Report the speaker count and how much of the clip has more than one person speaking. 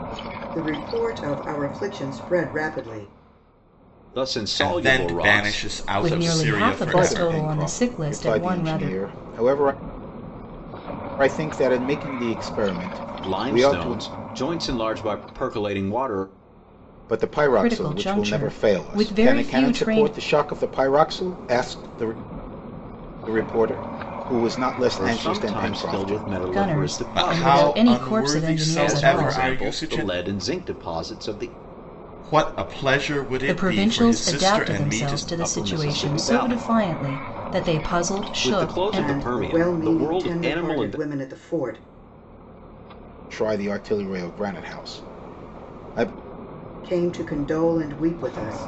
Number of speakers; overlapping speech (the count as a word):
five, about 38%